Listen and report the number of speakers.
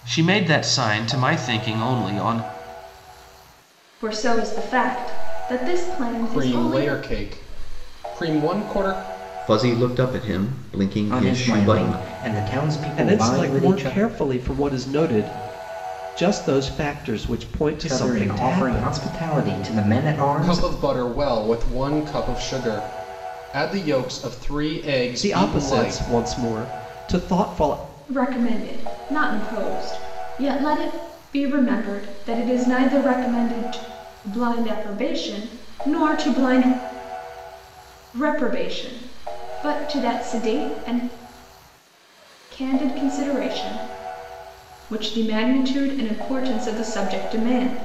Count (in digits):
6